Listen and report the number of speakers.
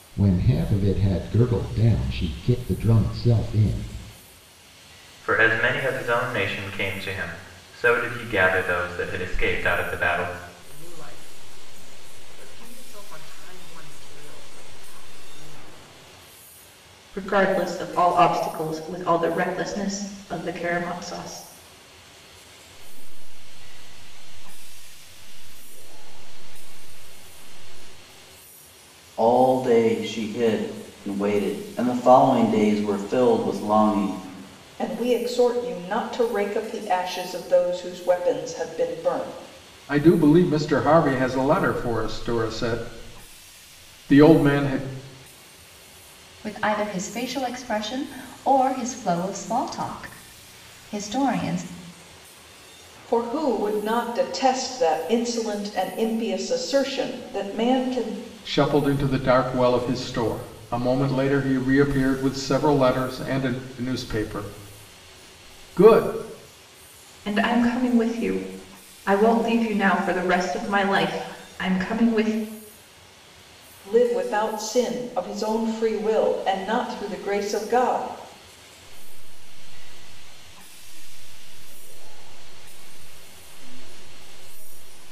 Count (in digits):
9